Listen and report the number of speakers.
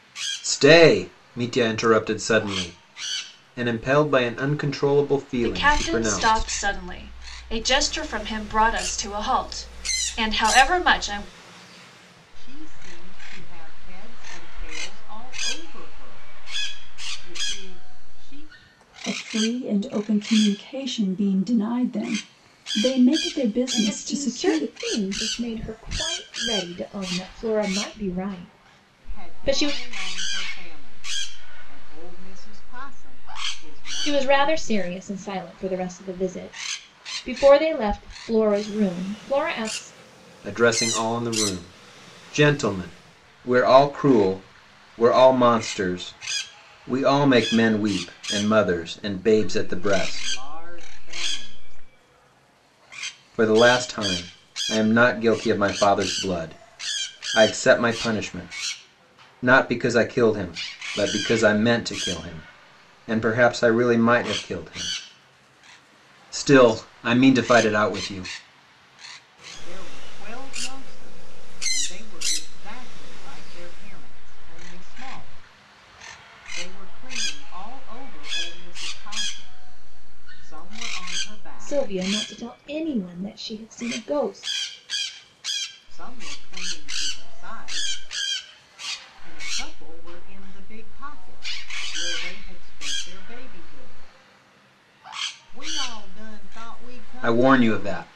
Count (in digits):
5